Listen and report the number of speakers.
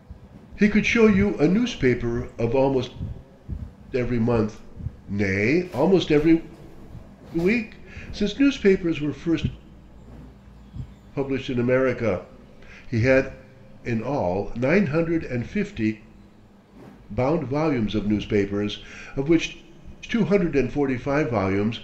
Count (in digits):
1